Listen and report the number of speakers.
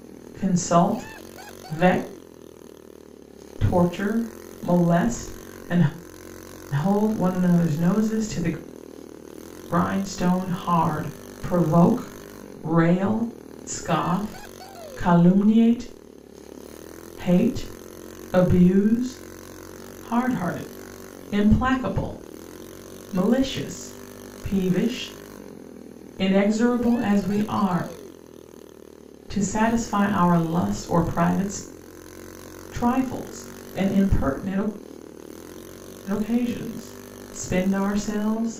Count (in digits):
1